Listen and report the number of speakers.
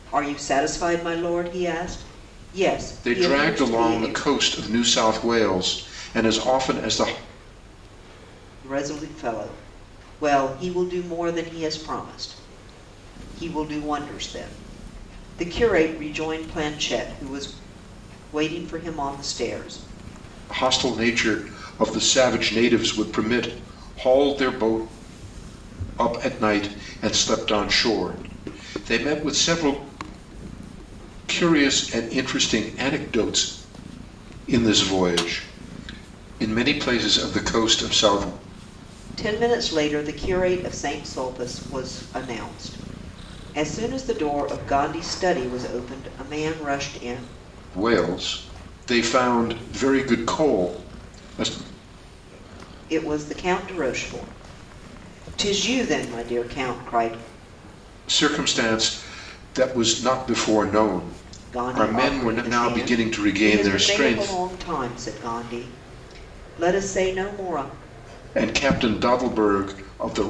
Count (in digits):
2